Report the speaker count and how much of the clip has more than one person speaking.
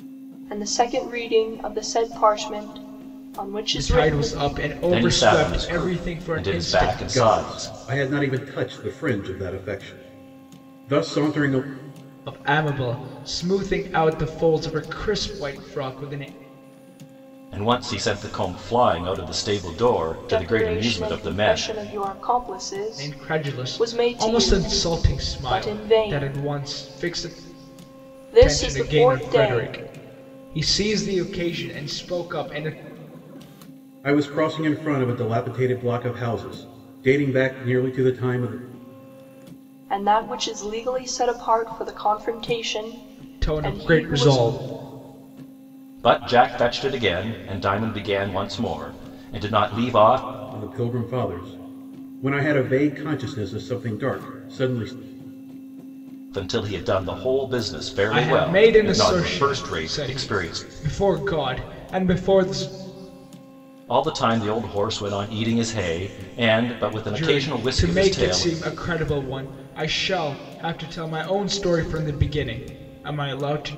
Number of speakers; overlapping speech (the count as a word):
four, about 20%